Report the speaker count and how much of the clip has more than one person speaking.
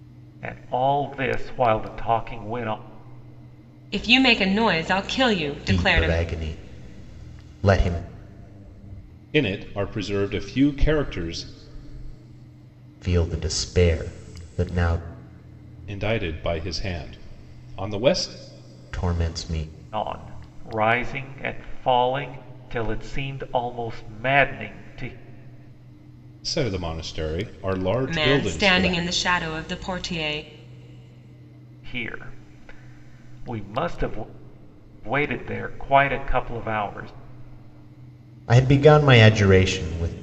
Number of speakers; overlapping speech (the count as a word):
four, about 4%